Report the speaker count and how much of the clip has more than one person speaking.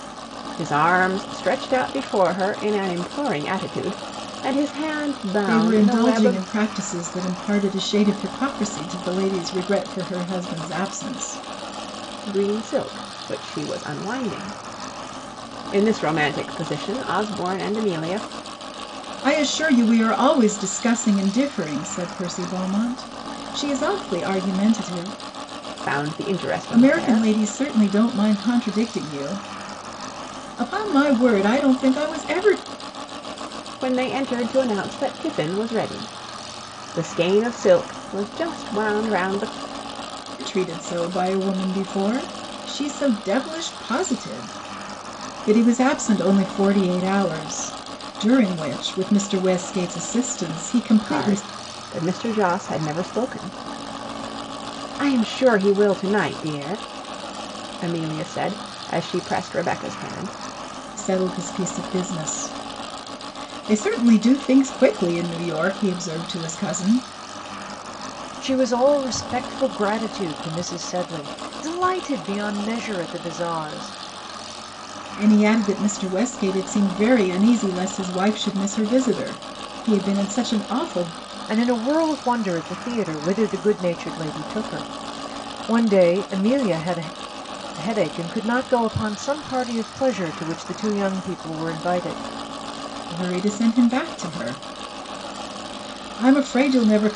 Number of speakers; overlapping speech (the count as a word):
two, about 2%